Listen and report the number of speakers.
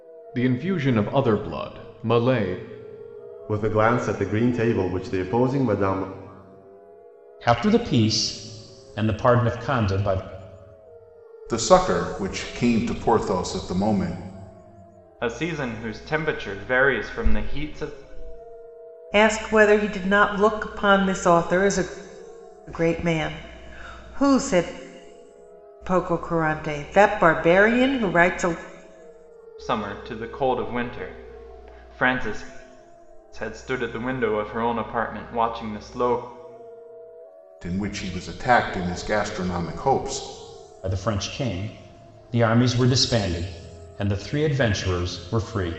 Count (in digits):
6